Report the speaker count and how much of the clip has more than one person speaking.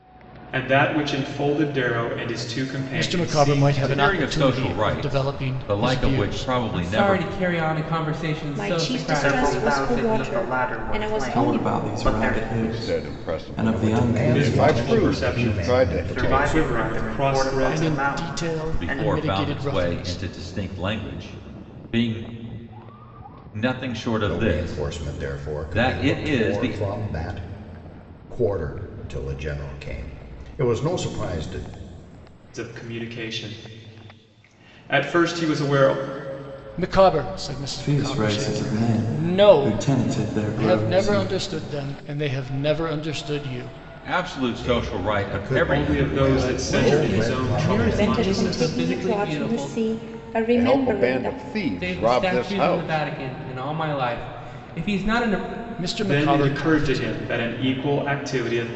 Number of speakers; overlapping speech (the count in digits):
9, about 51%